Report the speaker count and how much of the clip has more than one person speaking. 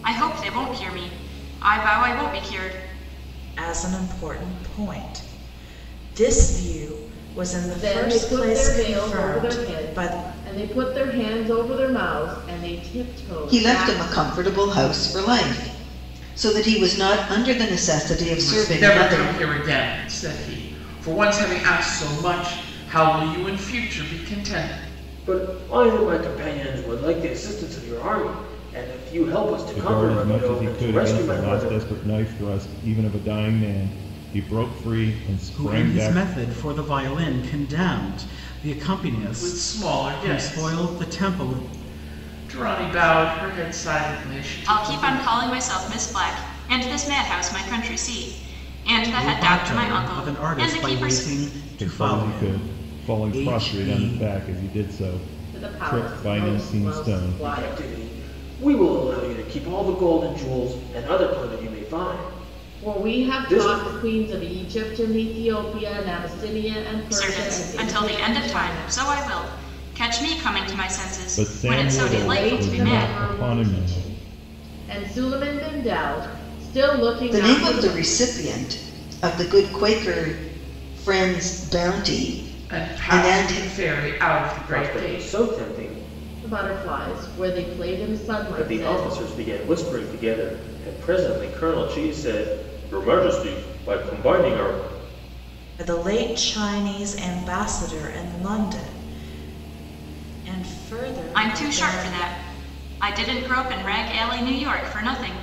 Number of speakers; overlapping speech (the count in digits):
8, about 26%